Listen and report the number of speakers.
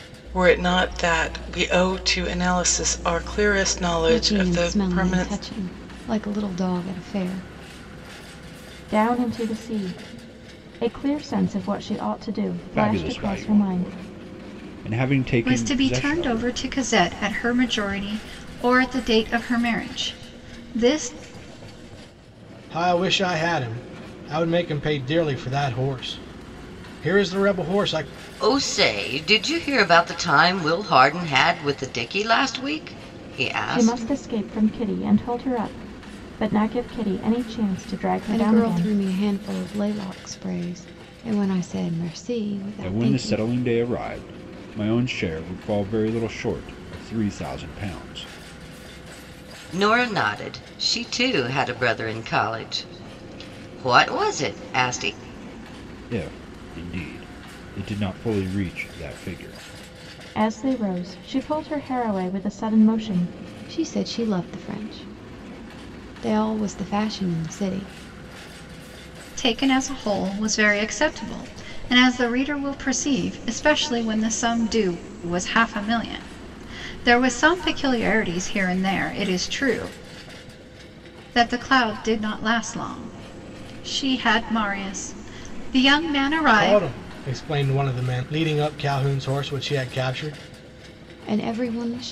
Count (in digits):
7